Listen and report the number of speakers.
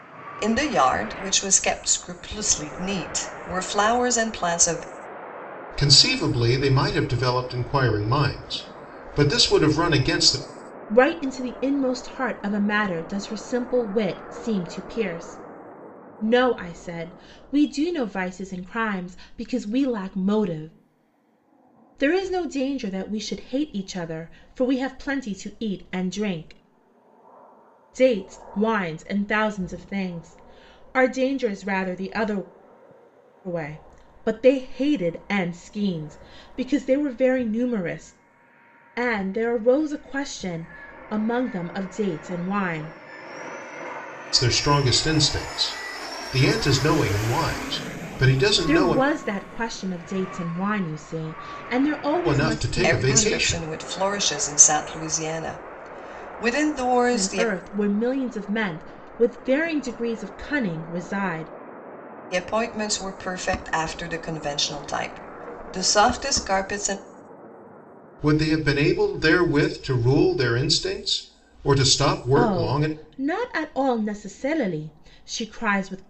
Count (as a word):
three